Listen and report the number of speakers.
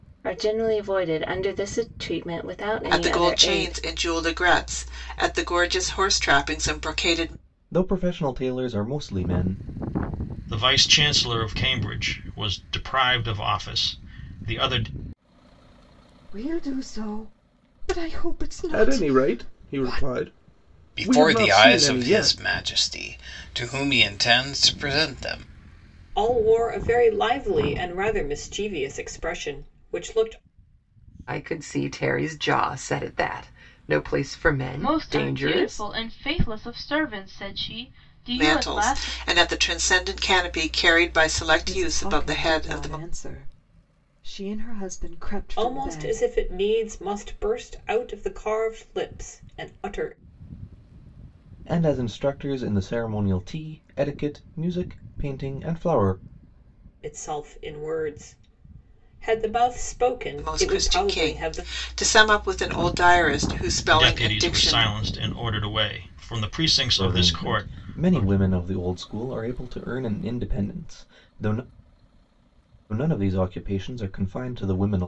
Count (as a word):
ten